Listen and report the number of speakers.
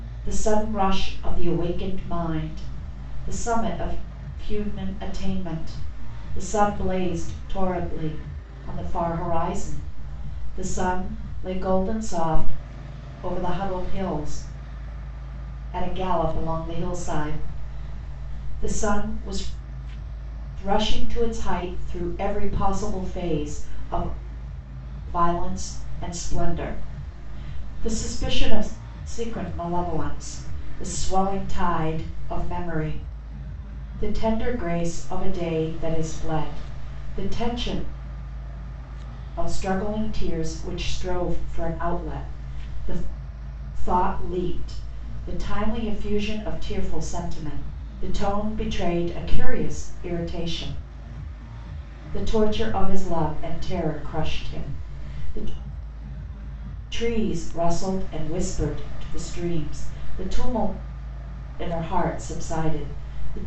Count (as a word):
one